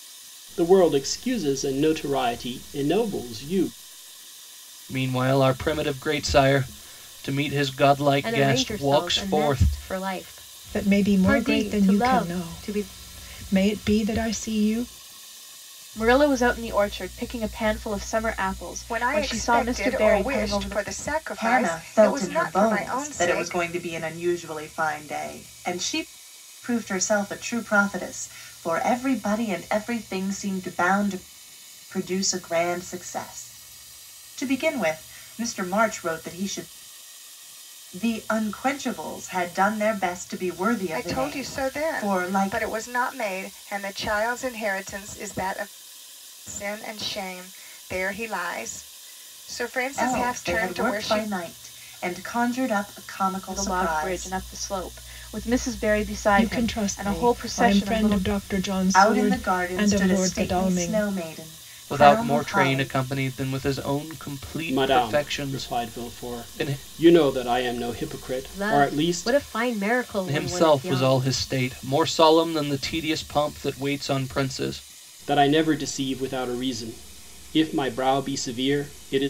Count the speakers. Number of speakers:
7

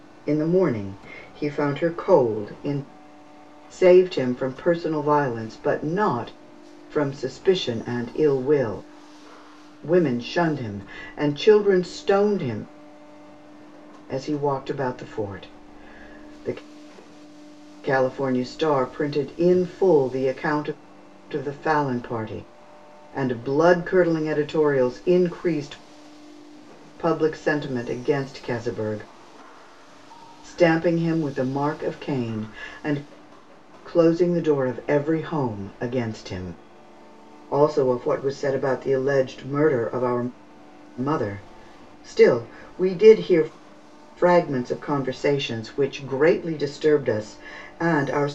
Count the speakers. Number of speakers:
1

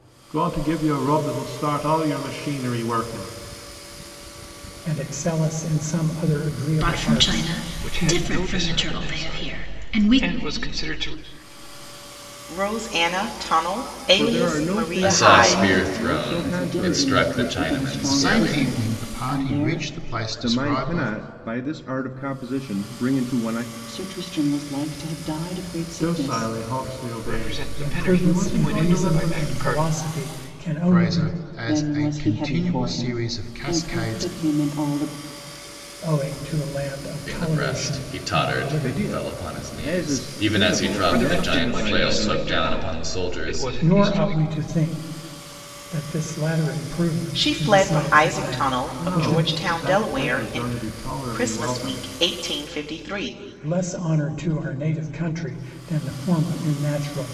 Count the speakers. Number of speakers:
9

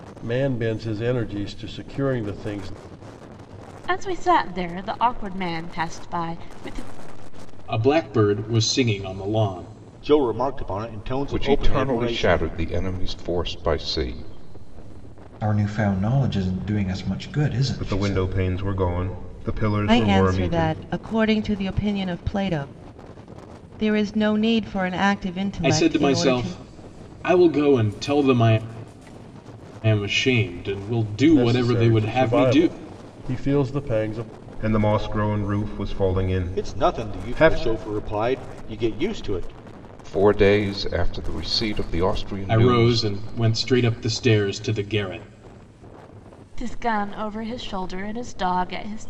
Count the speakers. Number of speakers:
8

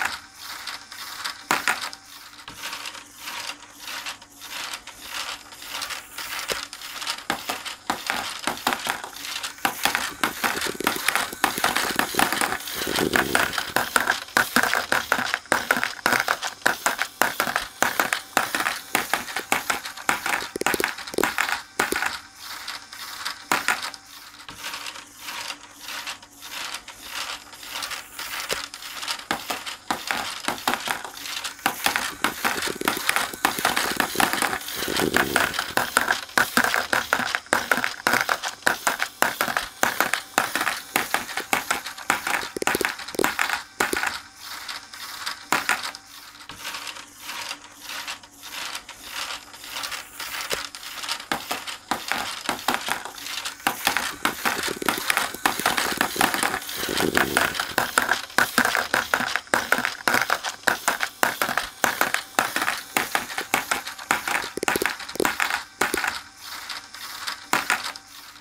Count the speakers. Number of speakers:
0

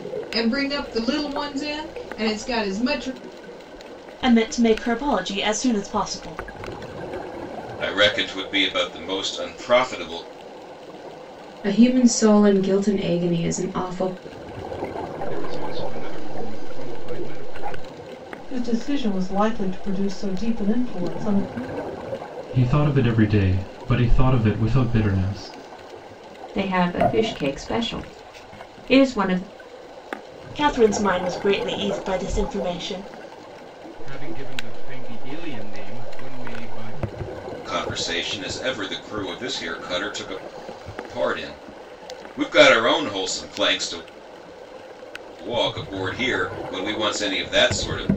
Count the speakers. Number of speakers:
8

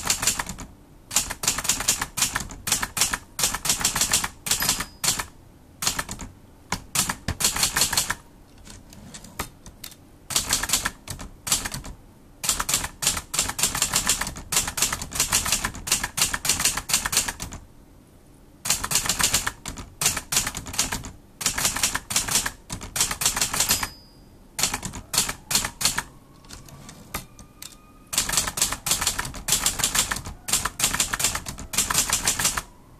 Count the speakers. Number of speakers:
0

